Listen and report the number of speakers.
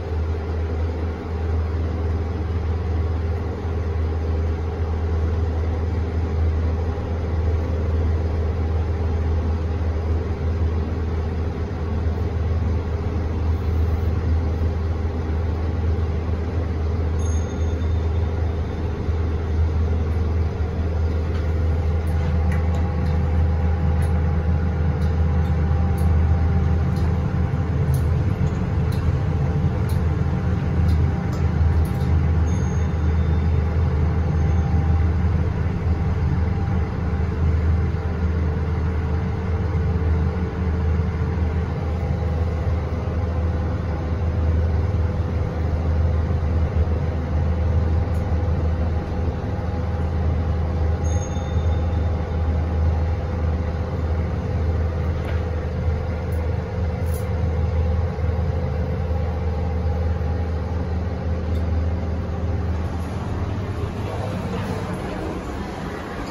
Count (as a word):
zero